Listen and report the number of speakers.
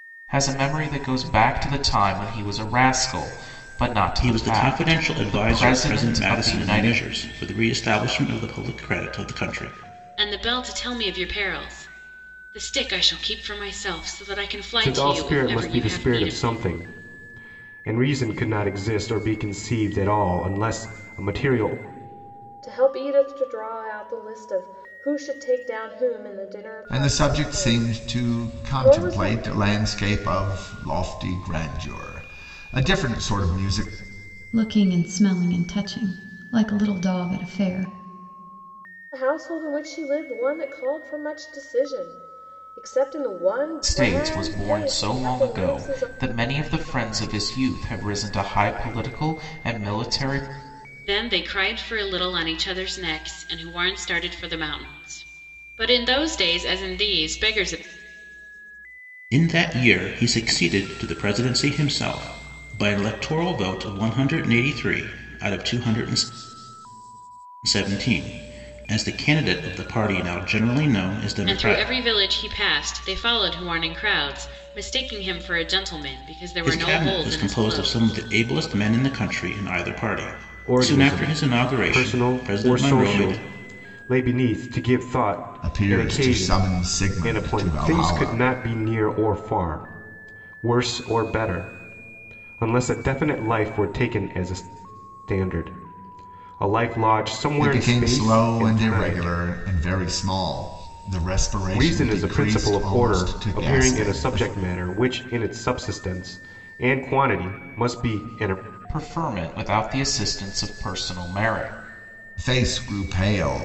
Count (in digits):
7